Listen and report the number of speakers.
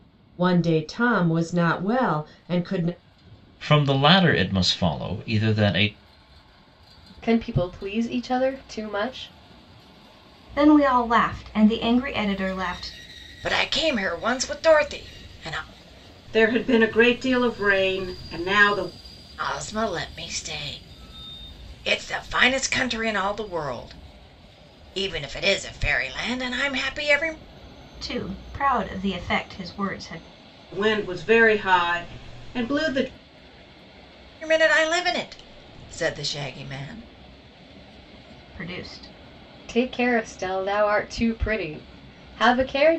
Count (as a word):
six